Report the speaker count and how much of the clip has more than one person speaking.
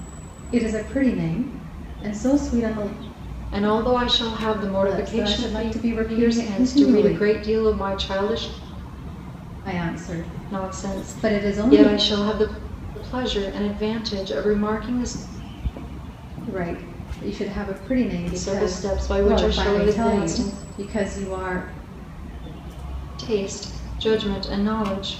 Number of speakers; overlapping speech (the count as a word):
two, about 22%